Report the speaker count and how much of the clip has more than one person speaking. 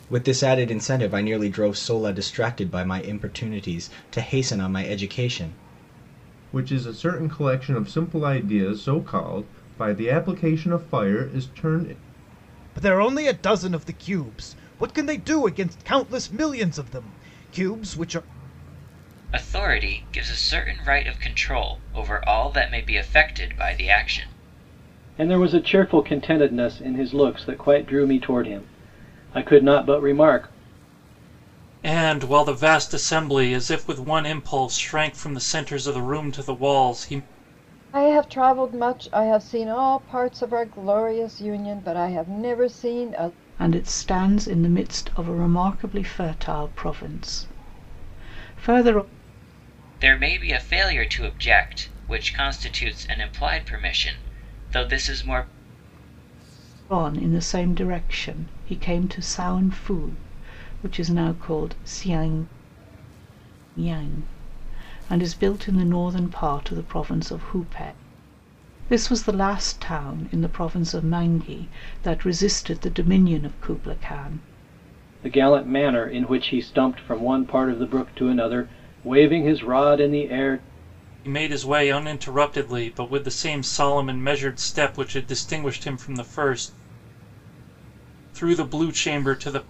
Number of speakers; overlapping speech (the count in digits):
8, no overlap